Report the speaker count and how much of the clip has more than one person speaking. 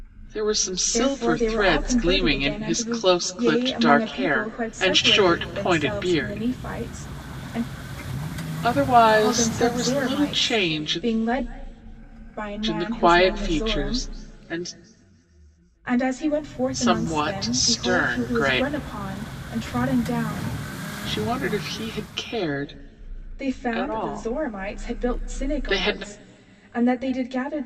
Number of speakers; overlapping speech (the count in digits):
2, about 47%